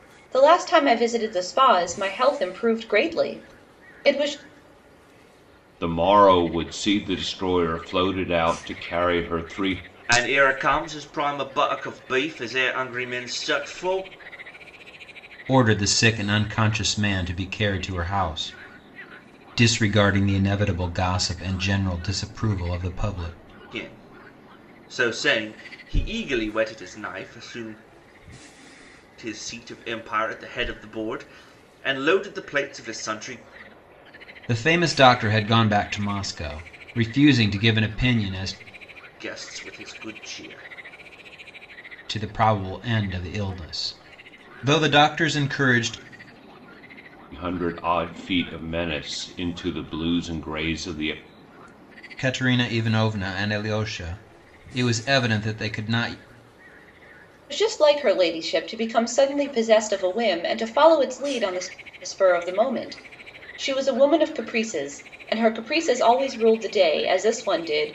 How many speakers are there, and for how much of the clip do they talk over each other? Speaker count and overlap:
4, no overlap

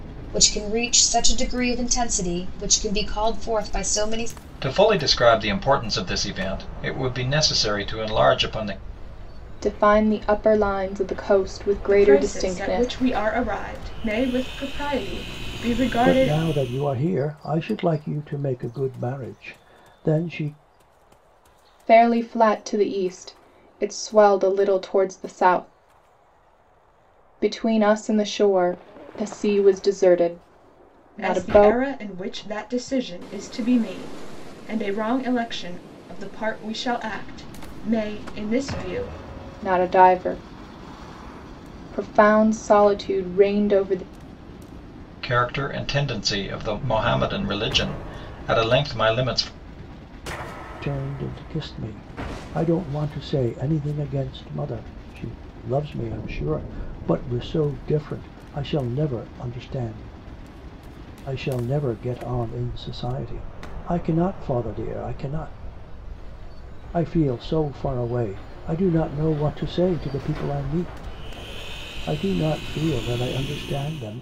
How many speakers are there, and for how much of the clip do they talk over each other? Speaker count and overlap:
5, about 3%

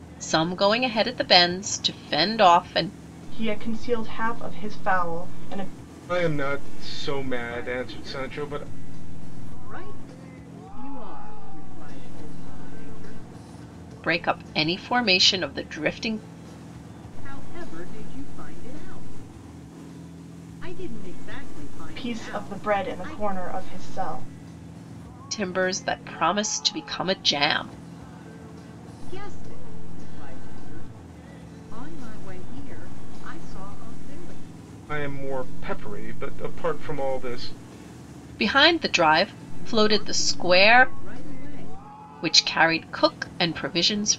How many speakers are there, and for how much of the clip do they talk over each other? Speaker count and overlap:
4, about 9%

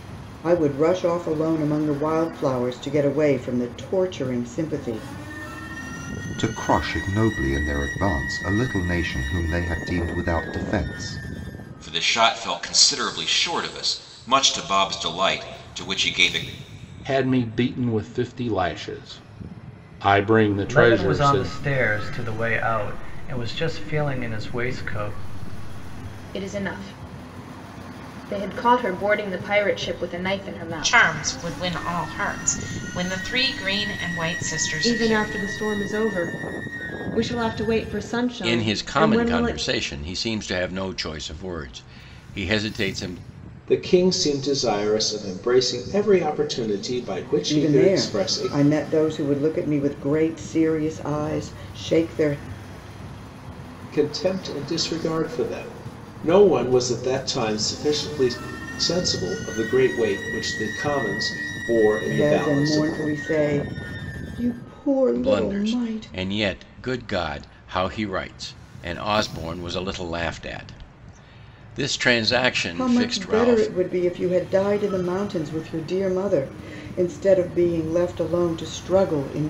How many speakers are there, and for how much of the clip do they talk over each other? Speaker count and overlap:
10, about 9%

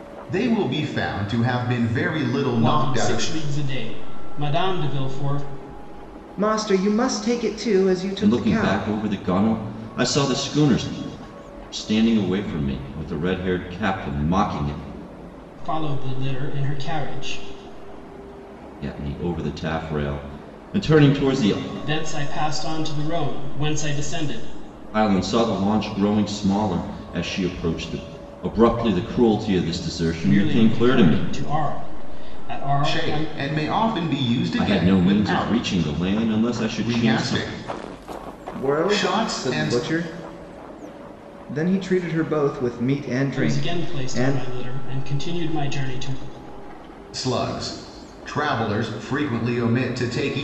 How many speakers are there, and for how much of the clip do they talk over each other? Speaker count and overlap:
4, about 14%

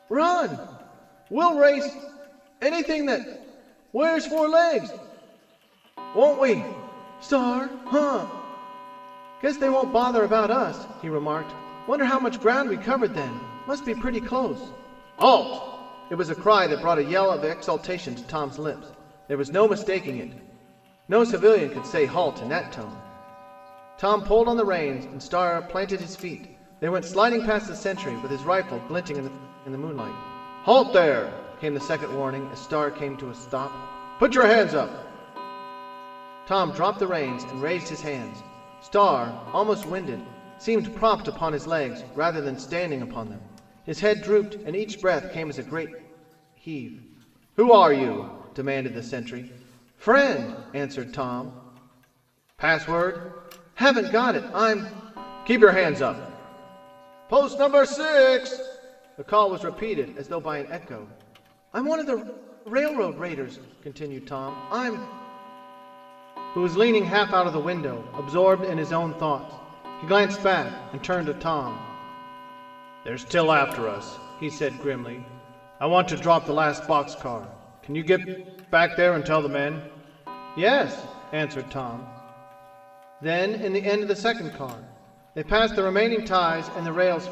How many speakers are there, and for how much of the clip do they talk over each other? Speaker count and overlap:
1, no overlap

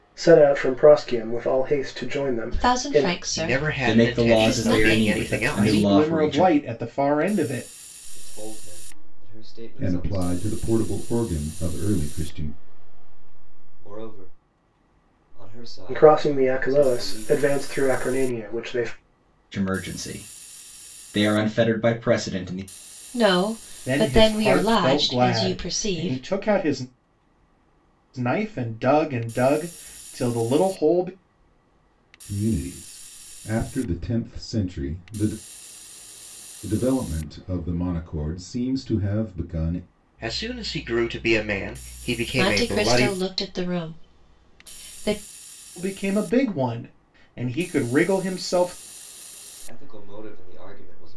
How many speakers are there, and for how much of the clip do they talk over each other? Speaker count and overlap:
7, about 23%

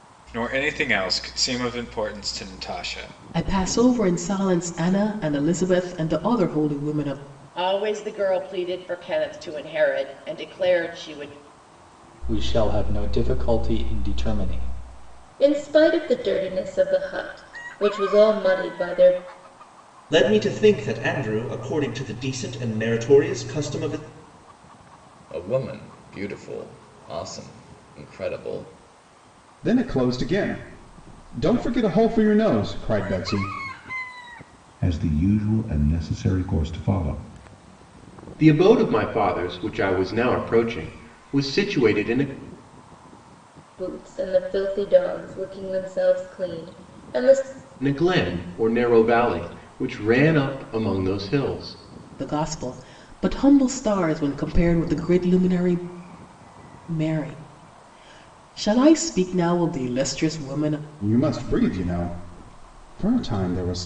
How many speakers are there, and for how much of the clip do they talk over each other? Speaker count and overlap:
10, no overlap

